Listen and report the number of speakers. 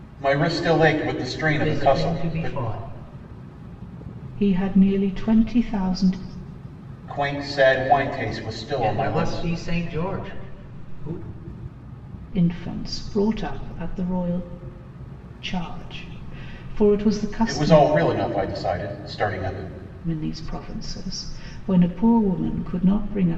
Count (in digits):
3